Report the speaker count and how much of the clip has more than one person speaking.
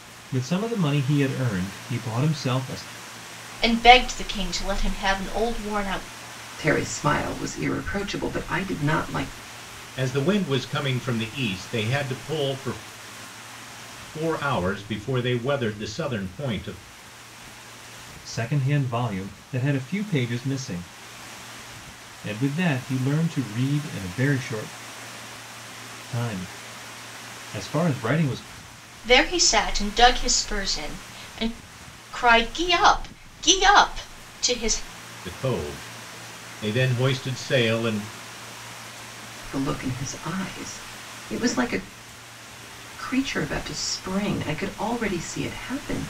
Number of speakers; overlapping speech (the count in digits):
4, no overlap